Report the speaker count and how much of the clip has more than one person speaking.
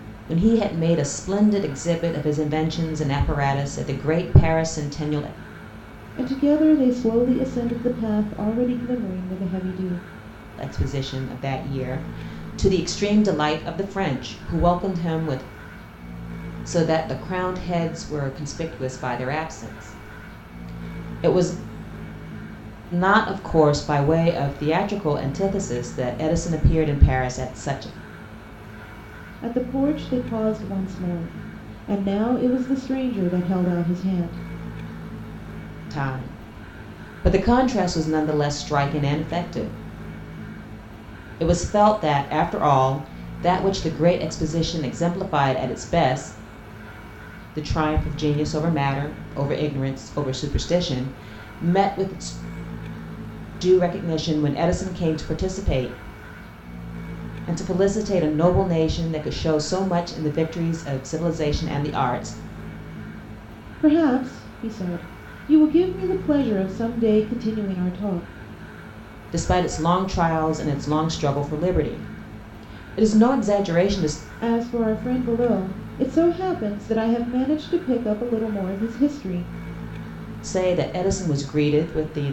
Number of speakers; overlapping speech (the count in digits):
2, no overlap